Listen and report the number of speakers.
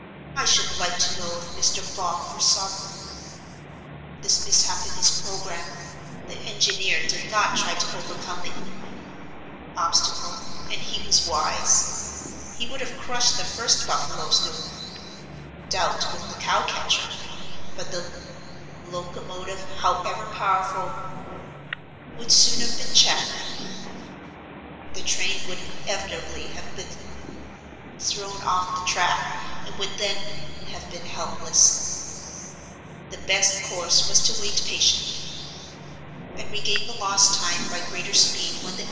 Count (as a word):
one